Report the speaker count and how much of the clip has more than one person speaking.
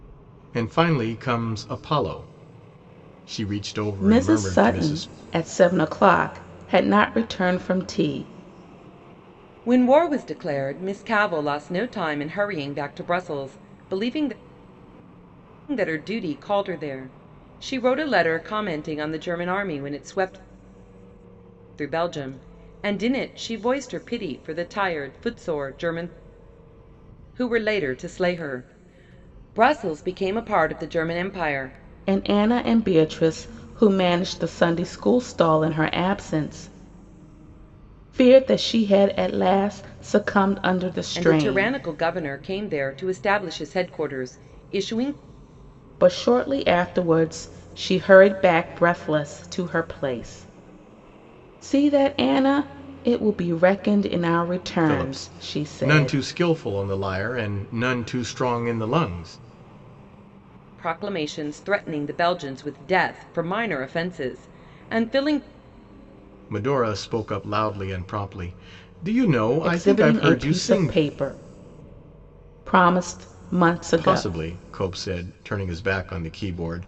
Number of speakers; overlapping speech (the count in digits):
3, about 6%